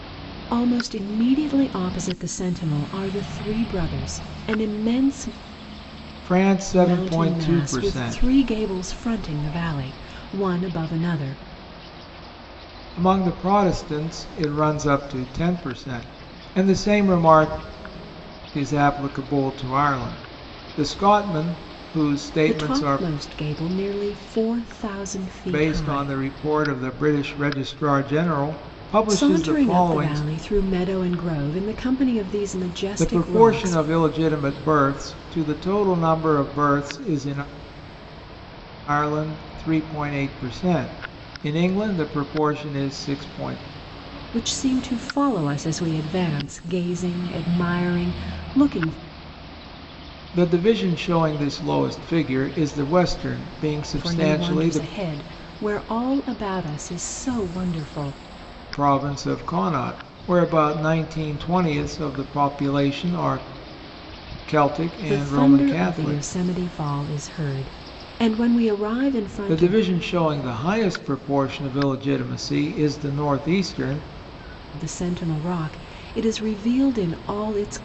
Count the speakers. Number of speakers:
two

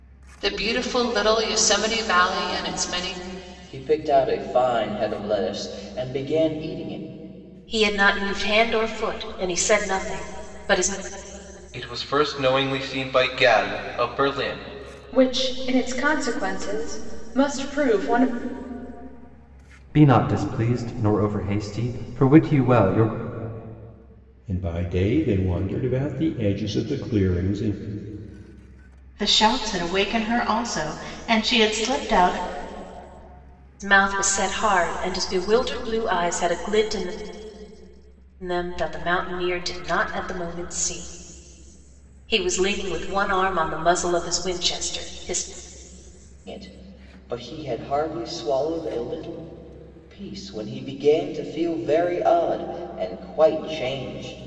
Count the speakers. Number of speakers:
eight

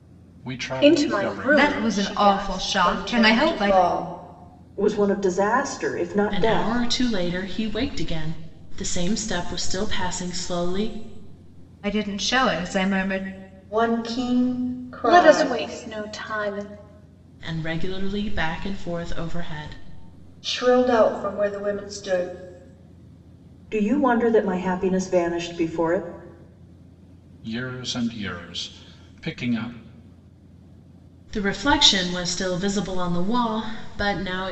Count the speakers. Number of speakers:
six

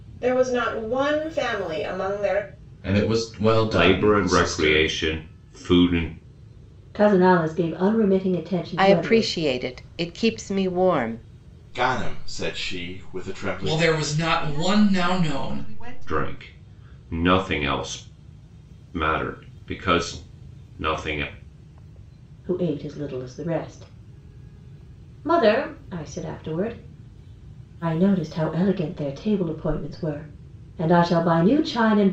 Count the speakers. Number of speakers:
eight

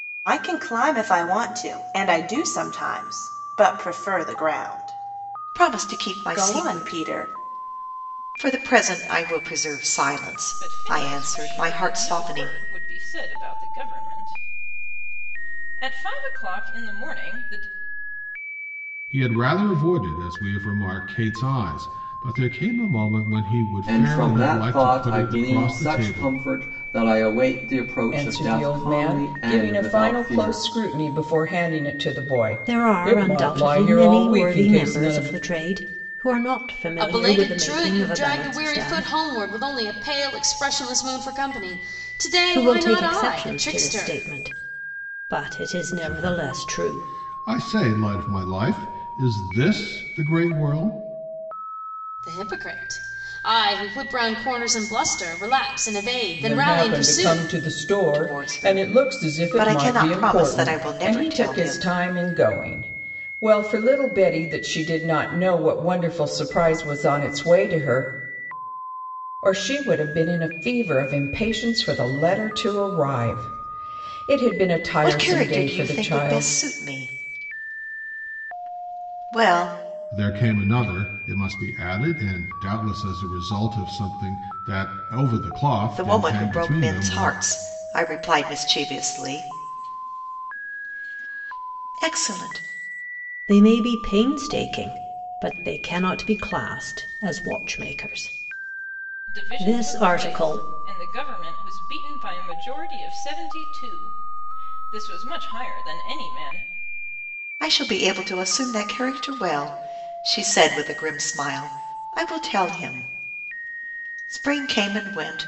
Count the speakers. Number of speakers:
eight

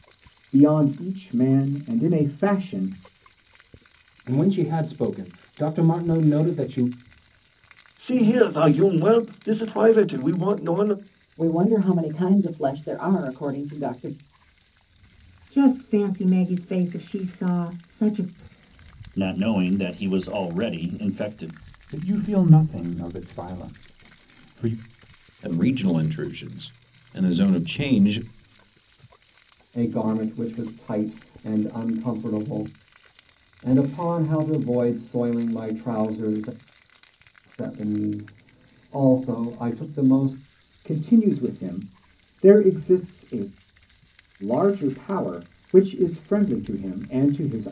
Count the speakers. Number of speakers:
nine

